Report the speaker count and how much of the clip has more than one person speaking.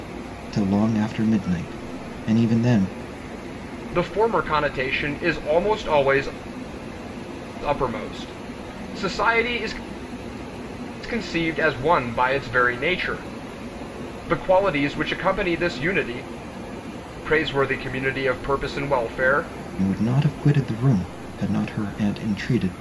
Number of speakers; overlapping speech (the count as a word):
two, no overlap